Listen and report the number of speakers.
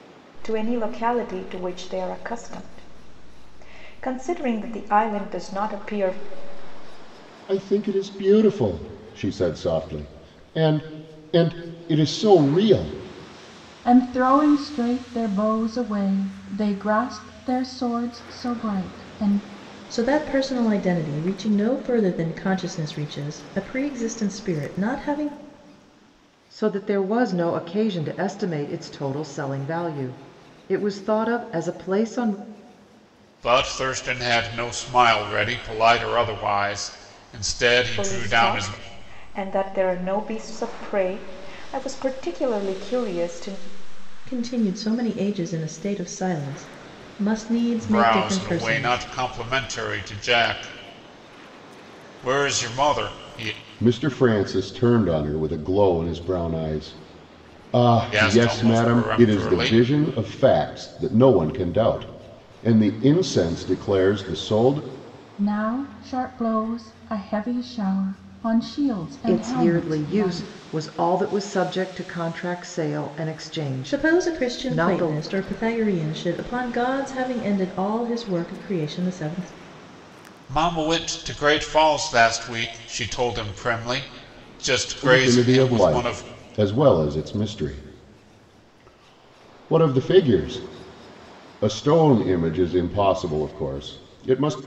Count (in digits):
6